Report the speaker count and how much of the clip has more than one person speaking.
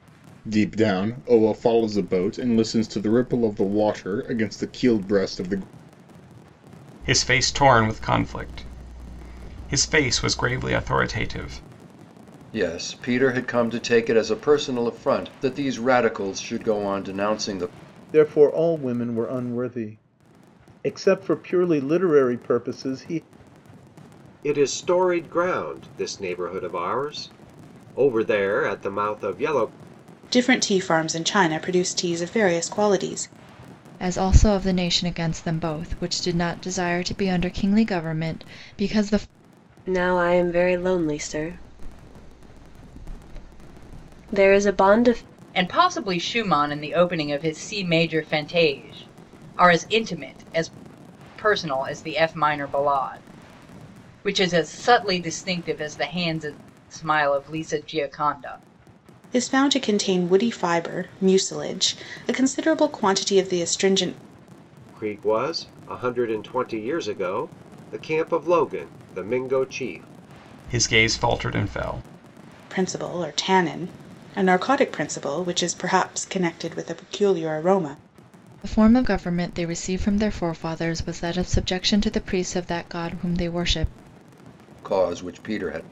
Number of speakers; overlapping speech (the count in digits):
9, no overlap